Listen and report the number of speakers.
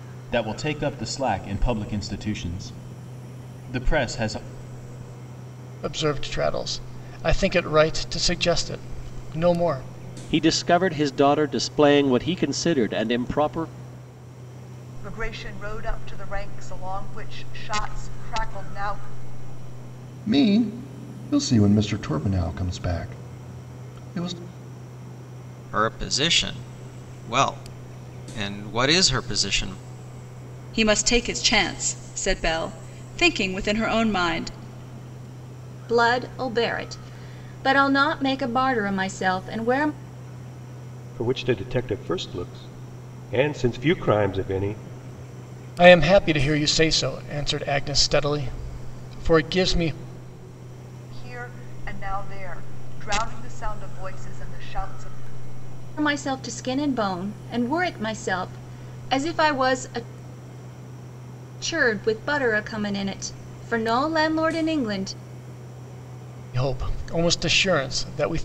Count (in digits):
9